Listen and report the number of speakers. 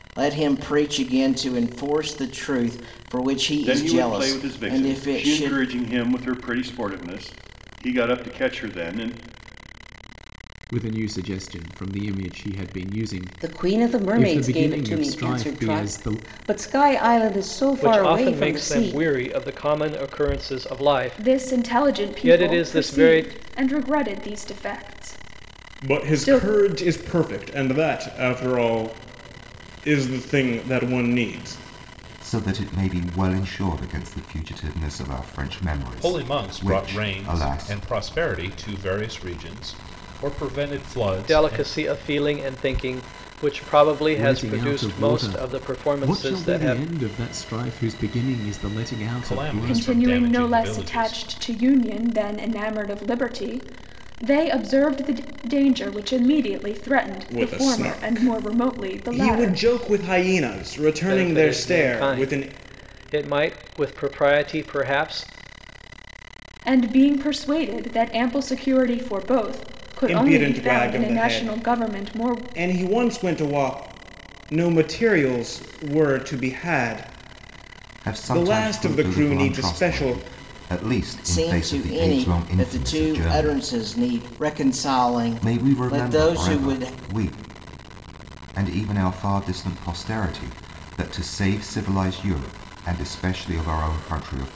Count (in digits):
9